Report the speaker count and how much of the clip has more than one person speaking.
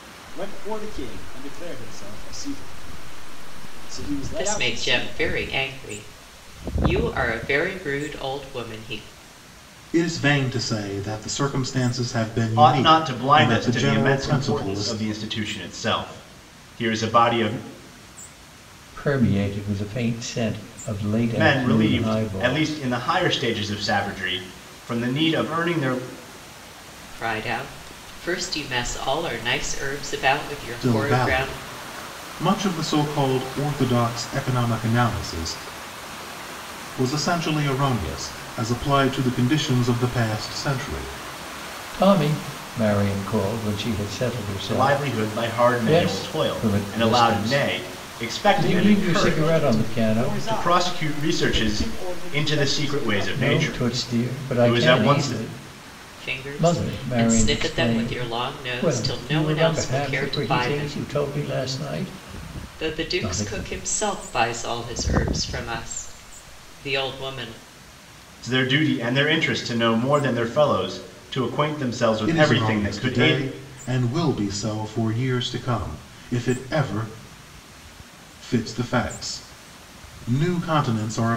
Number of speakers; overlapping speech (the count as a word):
five, about 28%